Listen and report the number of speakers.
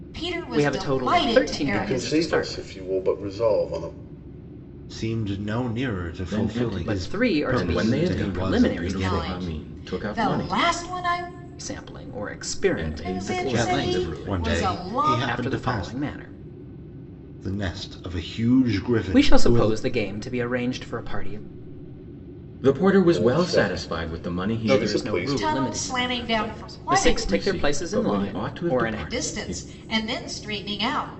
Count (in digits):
5